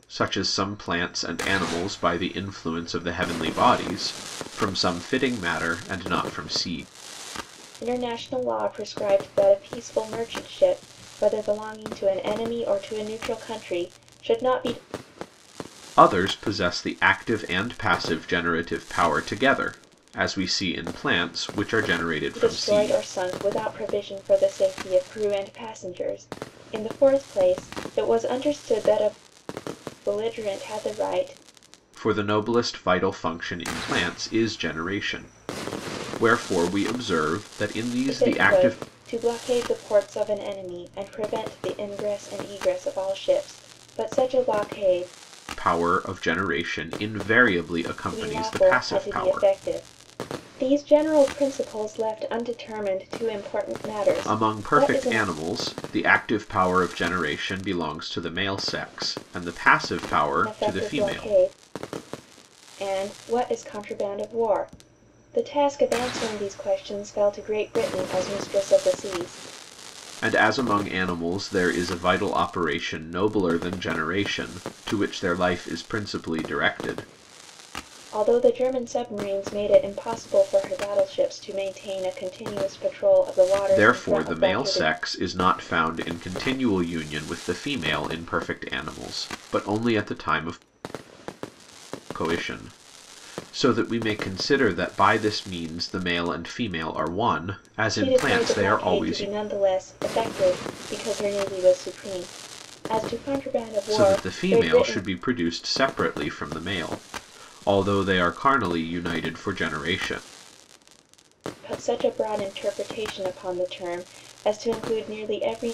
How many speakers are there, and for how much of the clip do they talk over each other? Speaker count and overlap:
2, about 8%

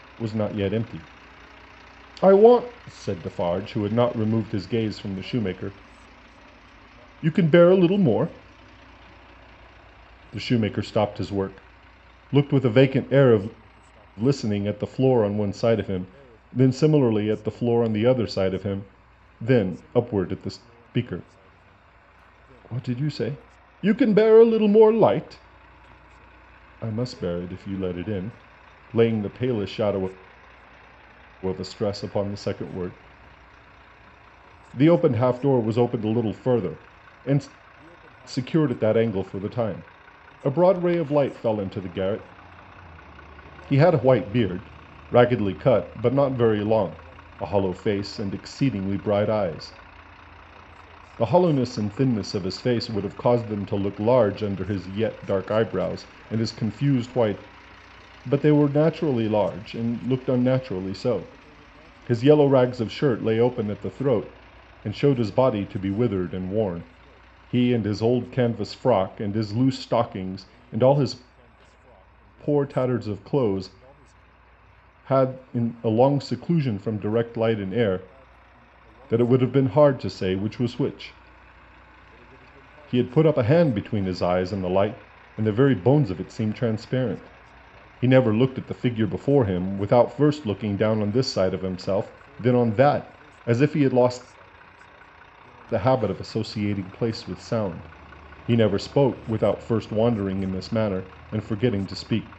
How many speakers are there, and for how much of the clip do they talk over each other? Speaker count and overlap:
1, no overlap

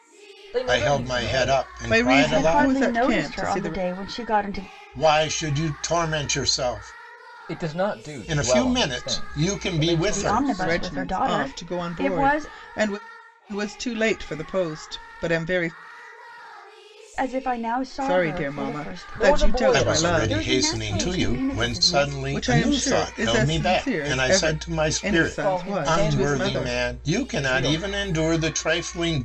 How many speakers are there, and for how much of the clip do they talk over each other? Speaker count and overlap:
4, about 56%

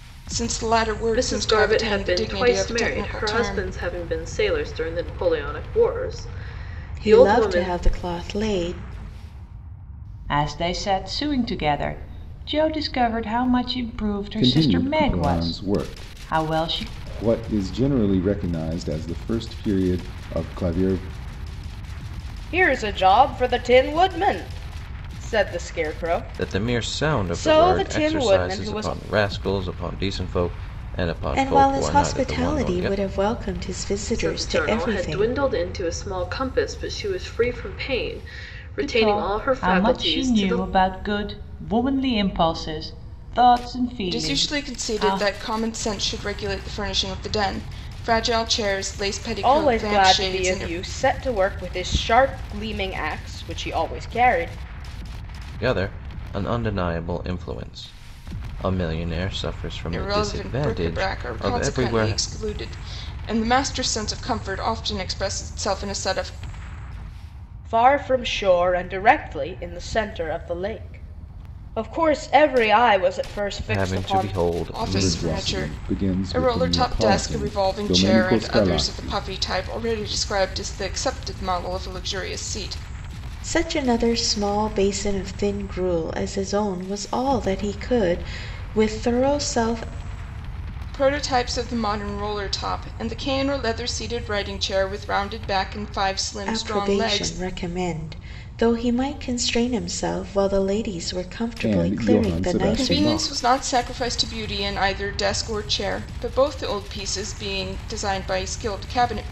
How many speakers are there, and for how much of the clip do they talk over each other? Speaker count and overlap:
7, about 23%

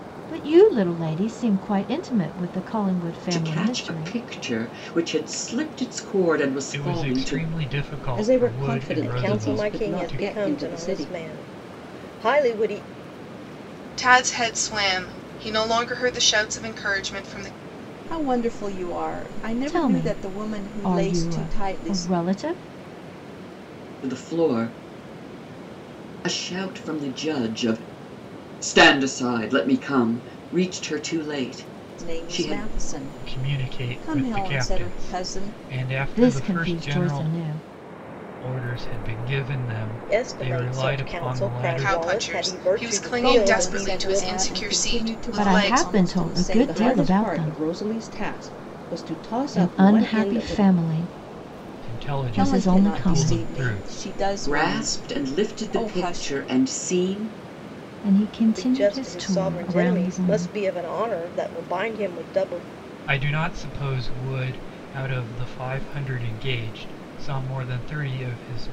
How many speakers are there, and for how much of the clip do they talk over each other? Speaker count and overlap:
7, about 38%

